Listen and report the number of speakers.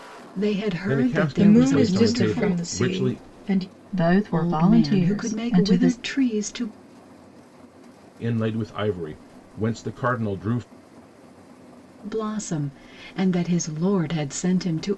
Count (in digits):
4